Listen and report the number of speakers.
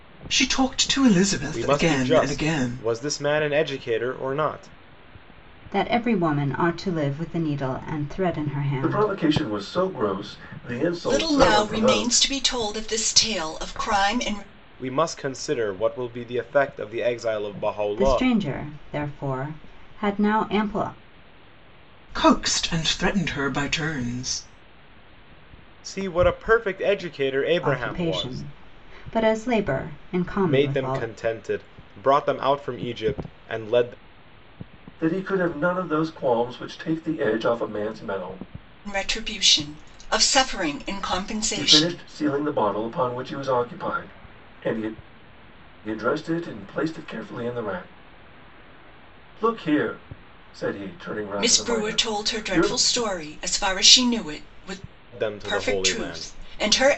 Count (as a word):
five